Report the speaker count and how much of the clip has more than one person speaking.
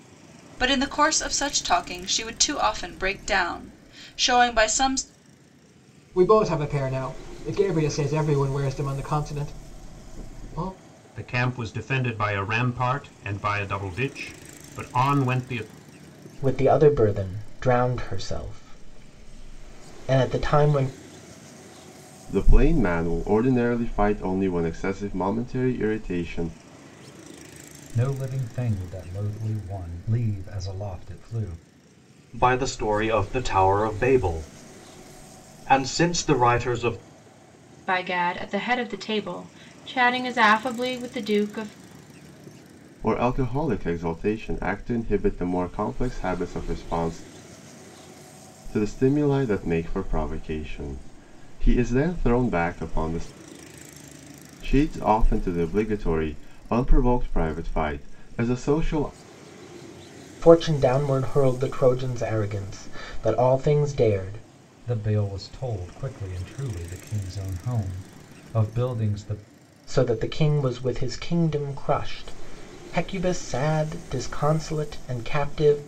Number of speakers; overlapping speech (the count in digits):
8, no overlap